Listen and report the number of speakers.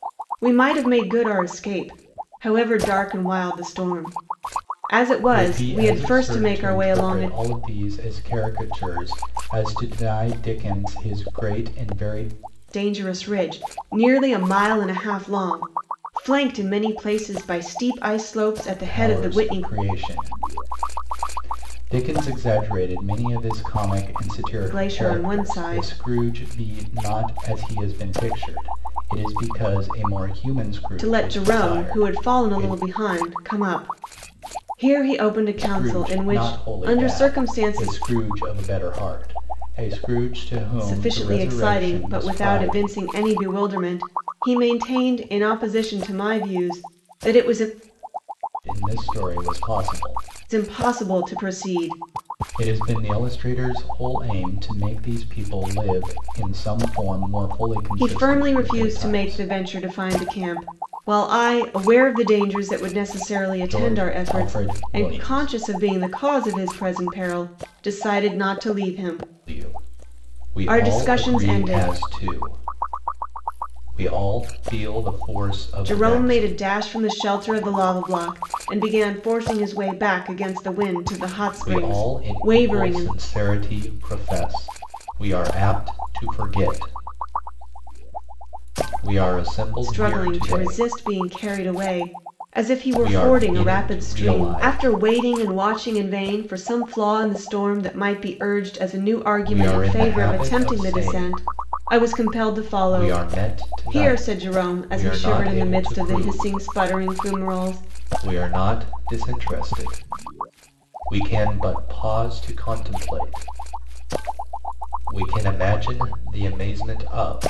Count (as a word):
two